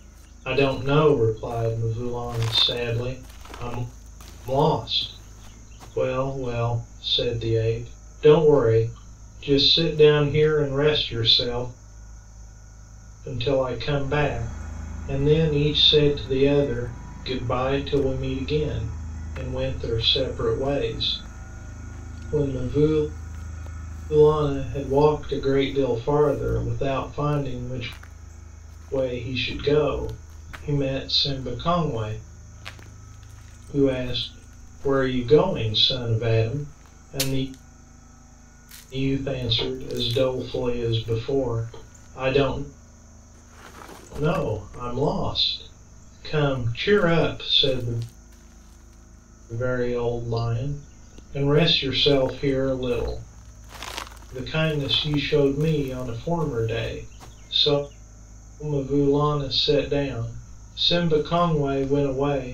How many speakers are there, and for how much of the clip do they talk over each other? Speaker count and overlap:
one, no overlap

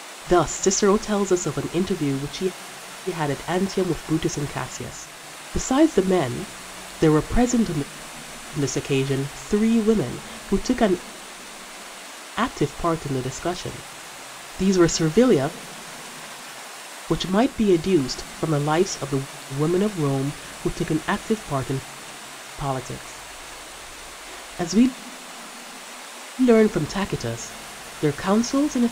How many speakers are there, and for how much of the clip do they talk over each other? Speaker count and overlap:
one, no overlap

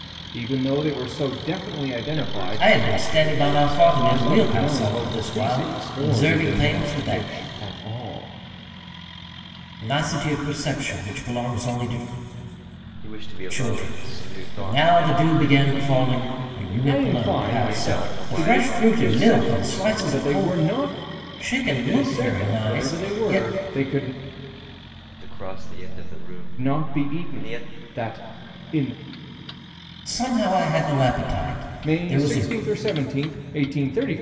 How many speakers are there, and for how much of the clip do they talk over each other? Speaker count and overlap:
three, about 44%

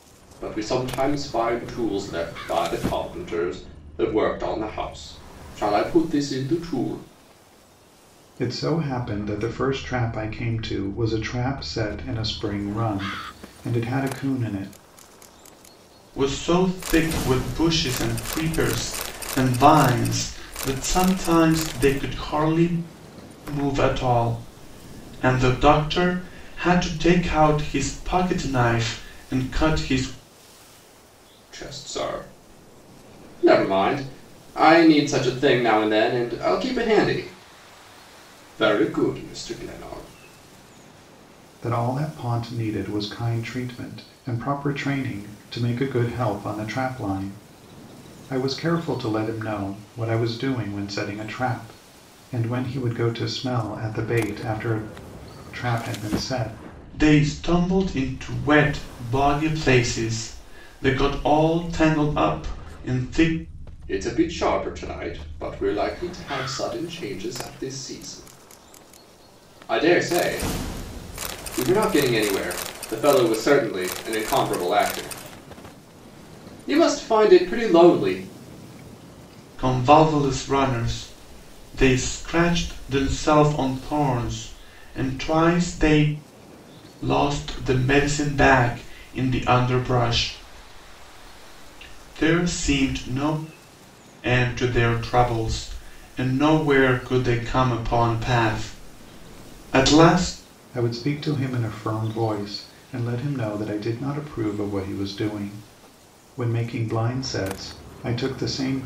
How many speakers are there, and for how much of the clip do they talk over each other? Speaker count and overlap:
three, no overlap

